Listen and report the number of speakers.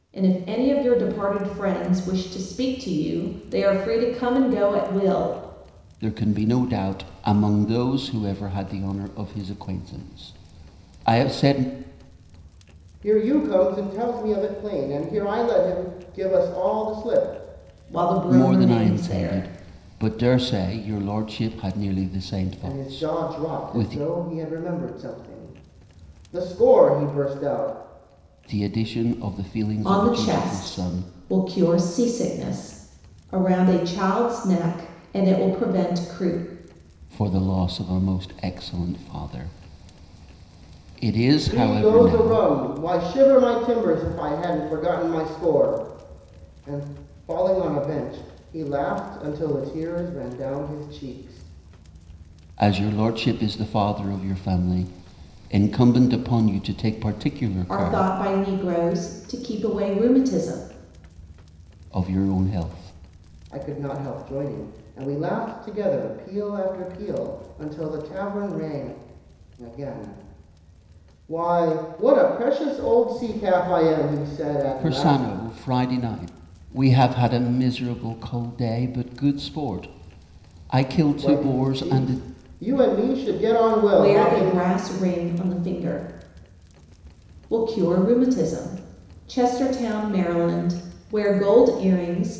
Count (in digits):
3